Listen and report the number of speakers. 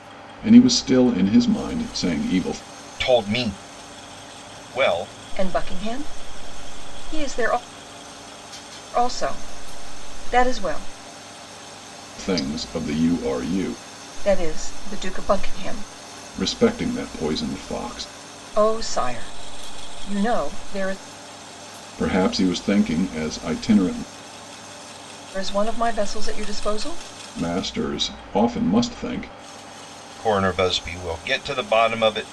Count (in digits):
3